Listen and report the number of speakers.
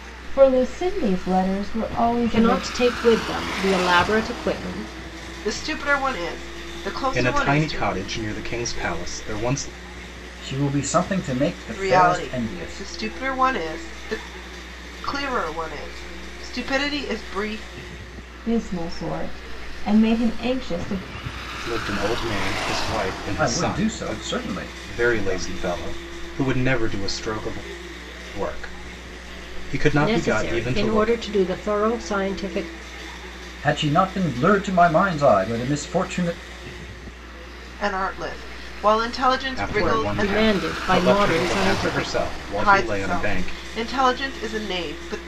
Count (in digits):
5